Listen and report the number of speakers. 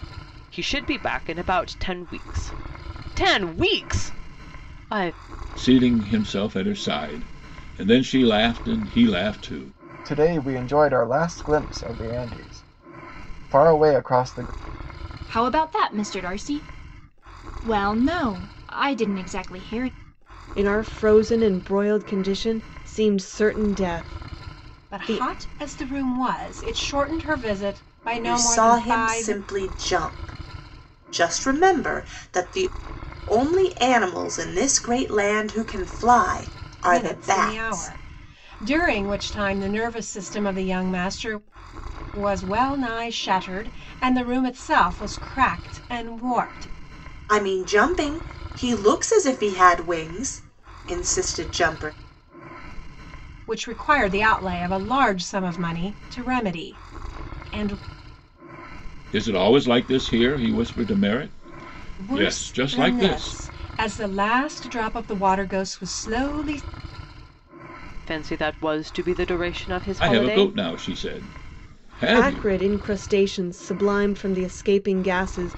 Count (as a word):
seven